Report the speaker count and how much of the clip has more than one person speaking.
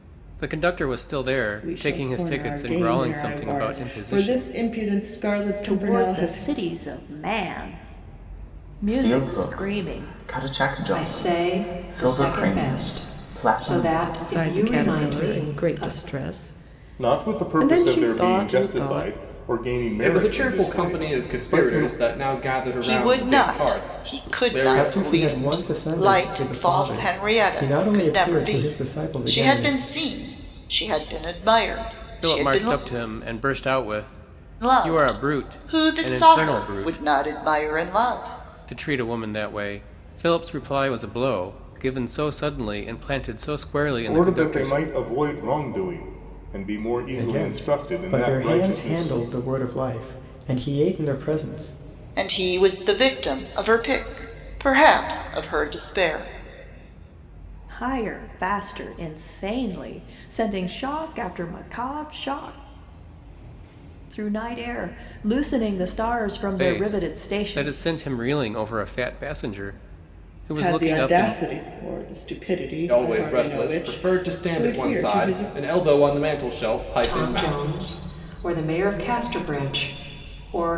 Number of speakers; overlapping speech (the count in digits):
10, about 40%